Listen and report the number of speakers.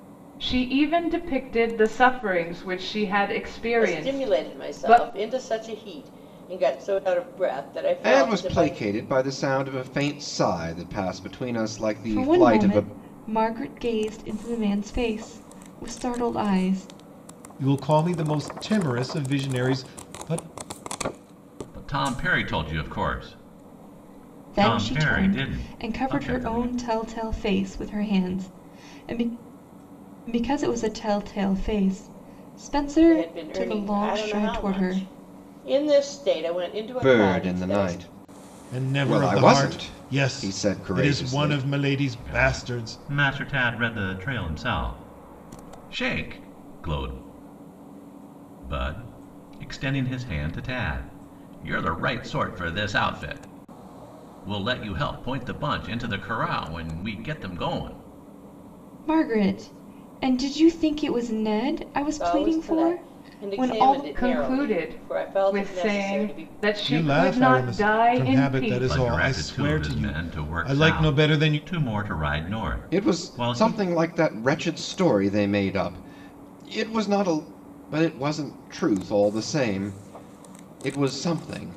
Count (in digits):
6